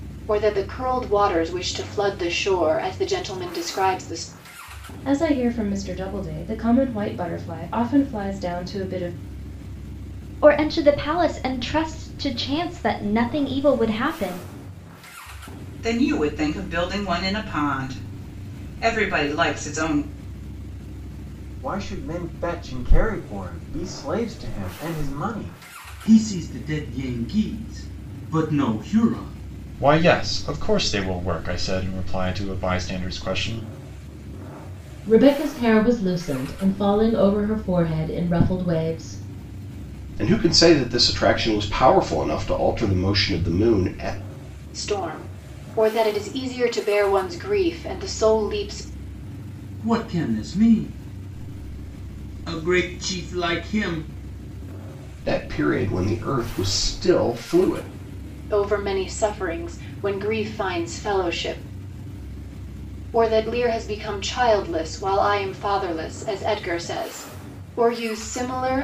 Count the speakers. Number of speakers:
9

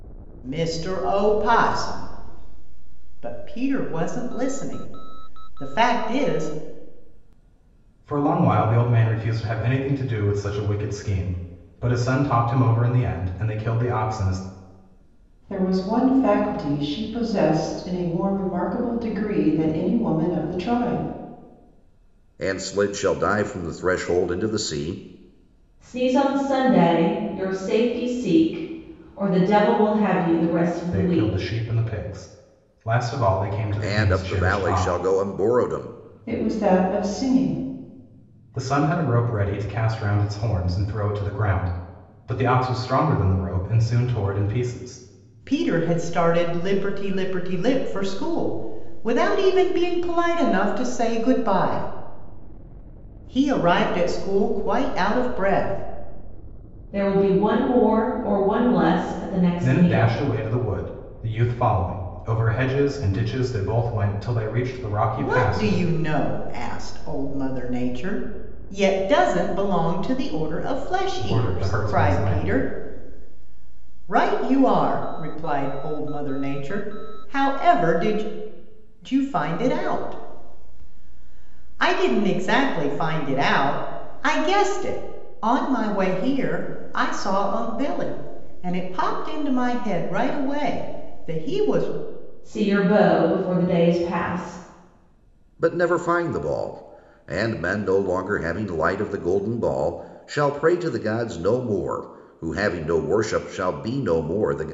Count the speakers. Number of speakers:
5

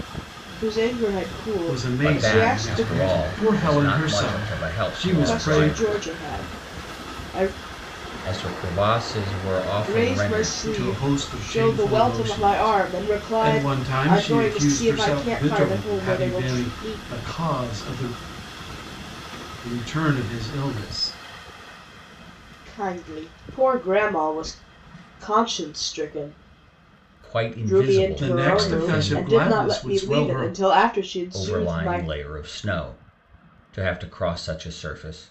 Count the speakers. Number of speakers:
3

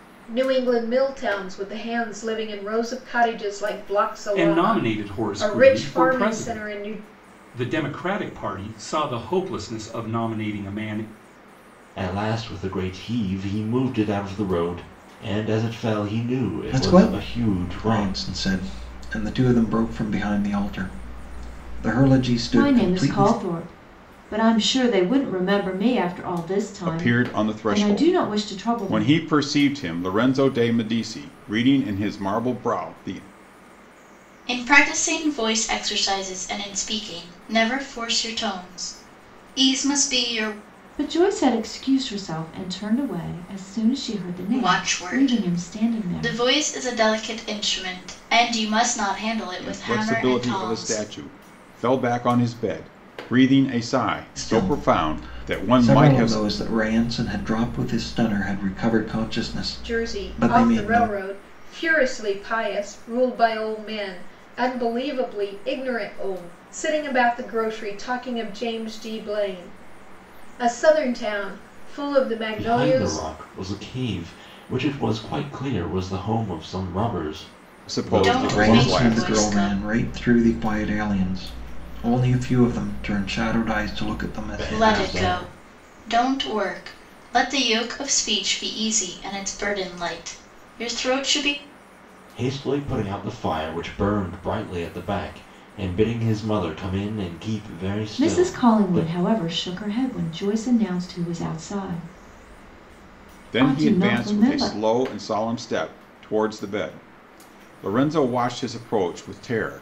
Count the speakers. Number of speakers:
7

